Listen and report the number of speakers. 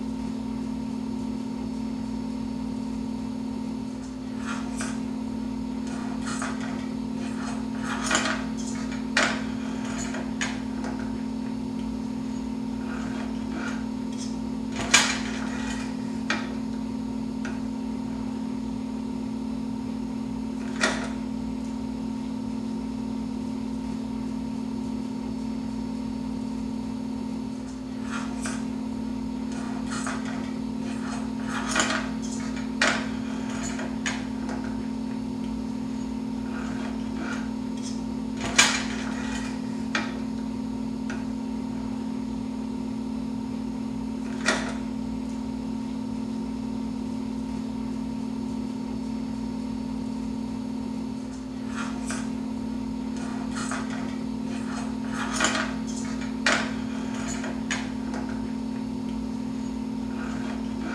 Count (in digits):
0